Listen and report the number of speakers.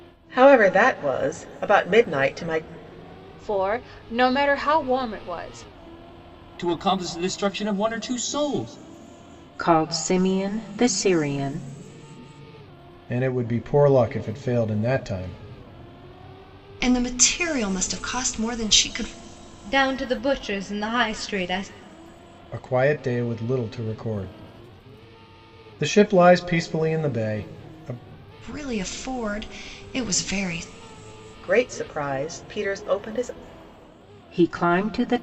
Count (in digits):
7